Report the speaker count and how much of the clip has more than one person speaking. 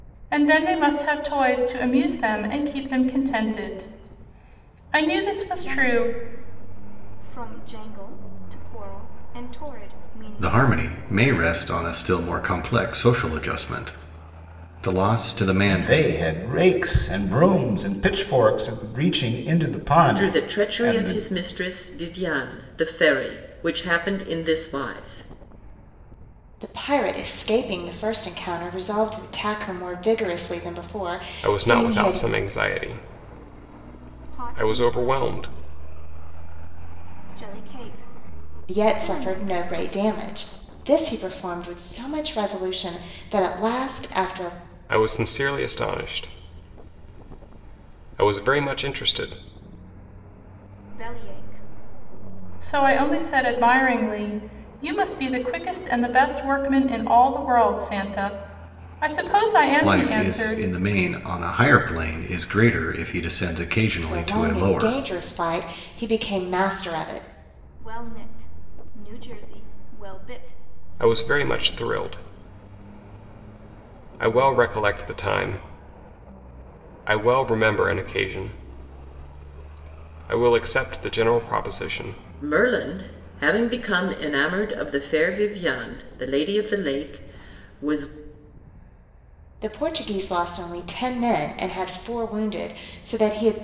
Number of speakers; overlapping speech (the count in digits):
7, about 10%